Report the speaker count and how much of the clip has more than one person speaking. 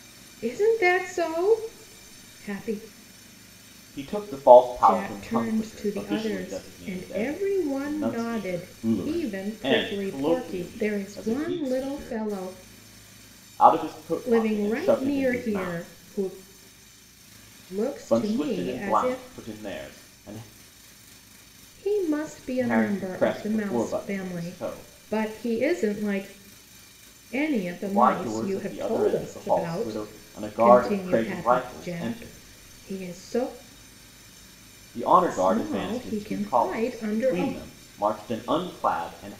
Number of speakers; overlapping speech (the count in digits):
2, about 48%